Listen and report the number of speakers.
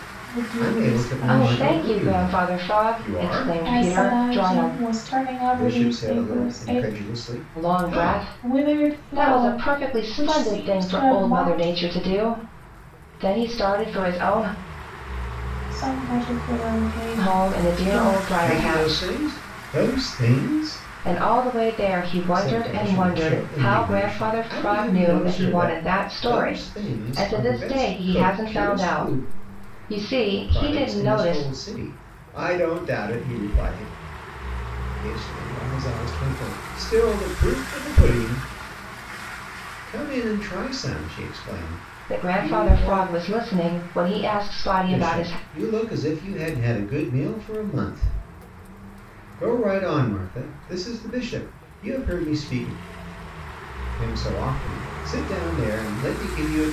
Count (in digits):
3